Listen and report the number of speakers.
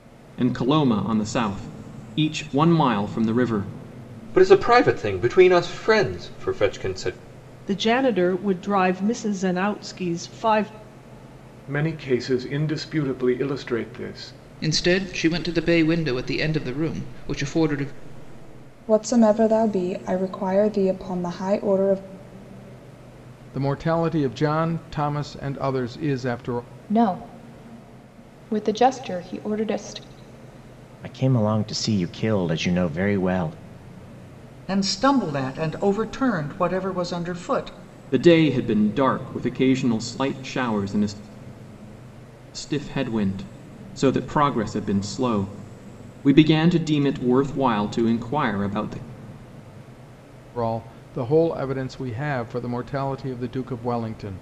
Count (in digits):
10